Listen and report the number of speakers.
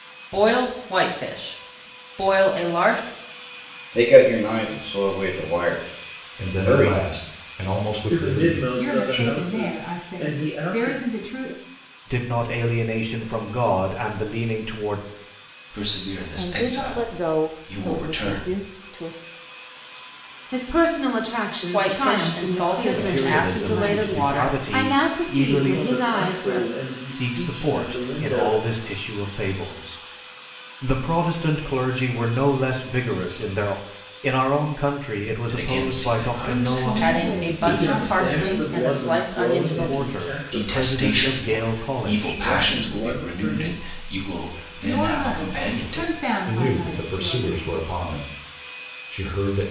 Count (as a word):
nine